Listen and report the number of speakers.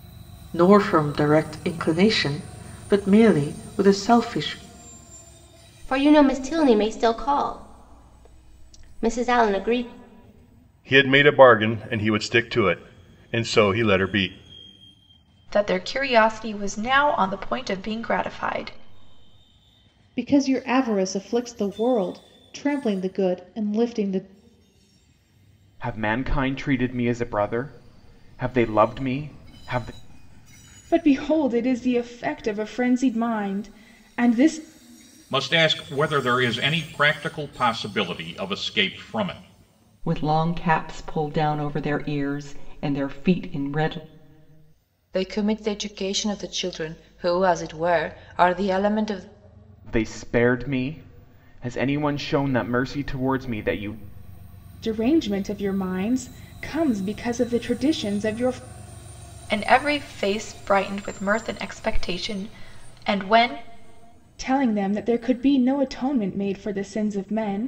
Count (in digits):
10